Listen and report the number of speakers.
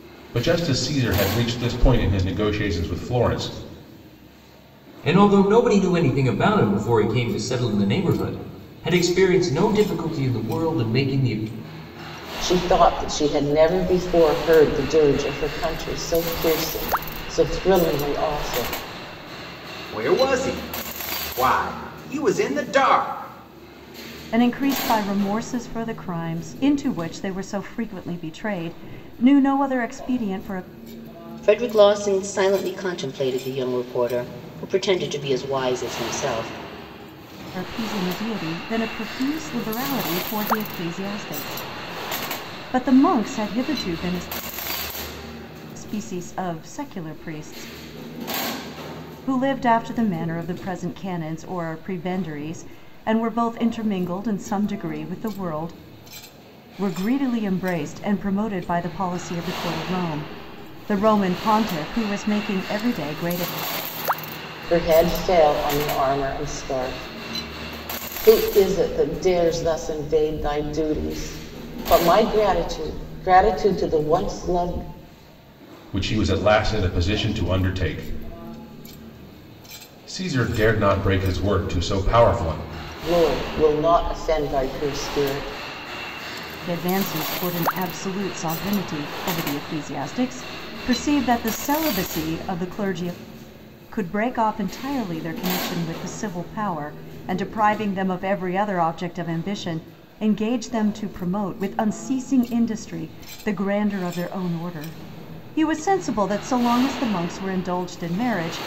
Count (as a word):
six